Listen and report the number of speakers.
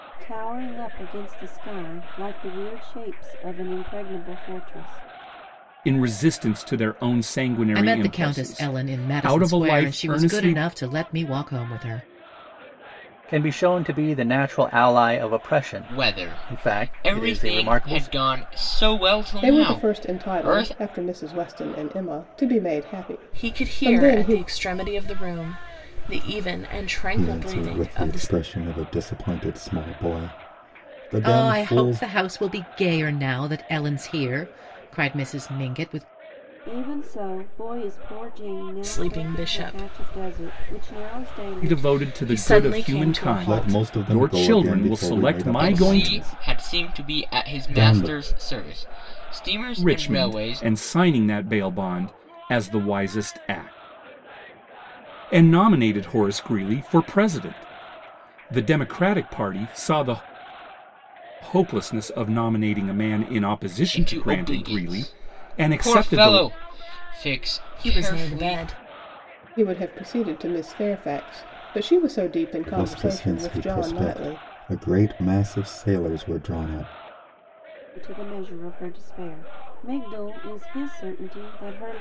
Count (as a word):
eight